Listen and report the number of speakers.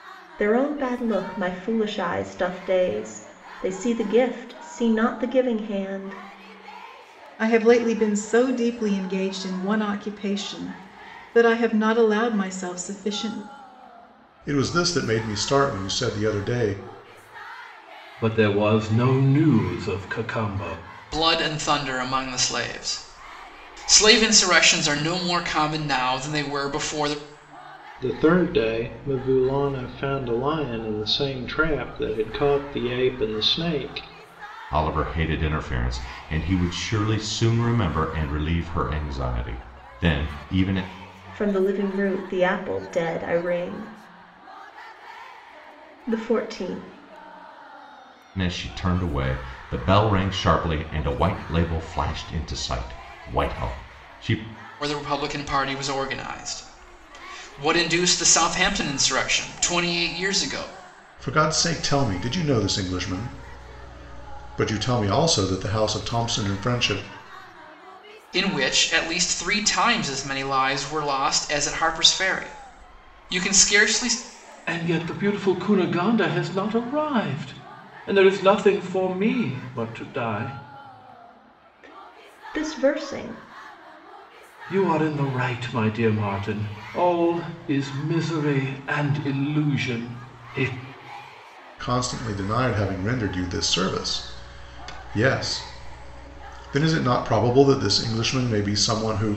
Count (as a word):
seven